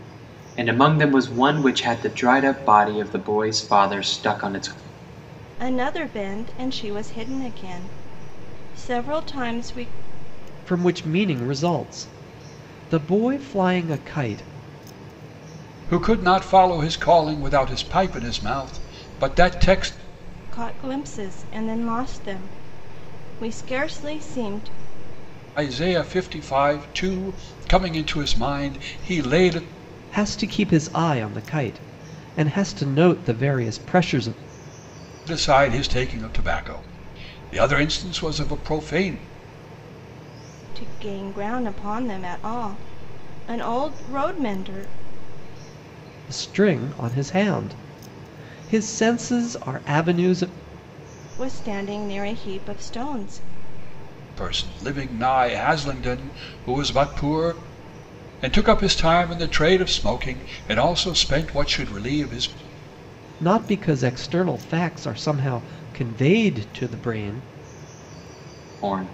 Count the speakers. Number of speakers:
4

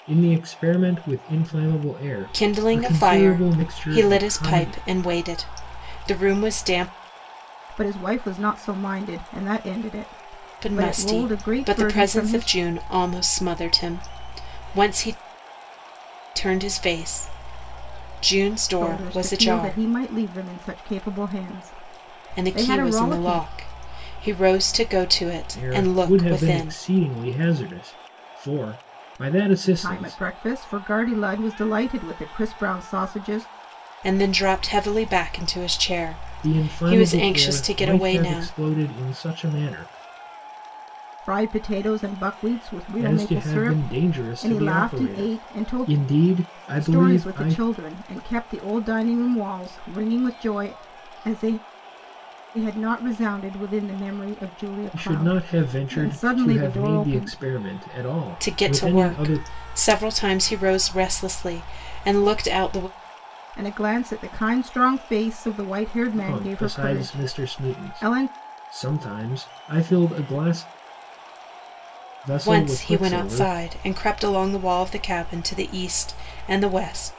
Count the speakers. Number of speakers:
3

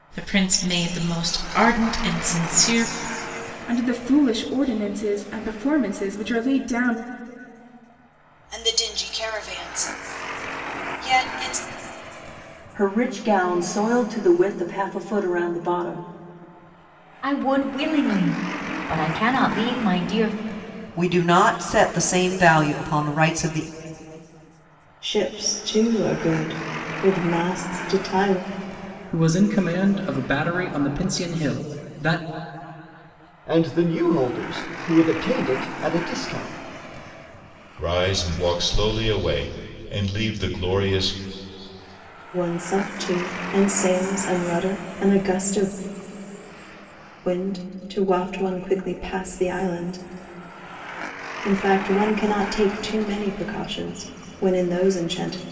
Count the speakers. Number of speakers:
10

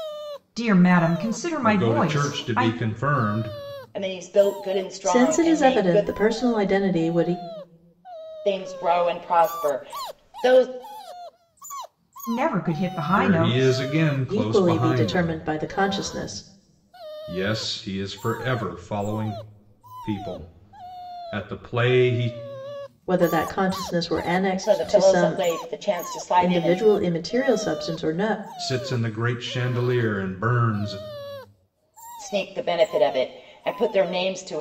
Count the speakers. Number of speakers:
4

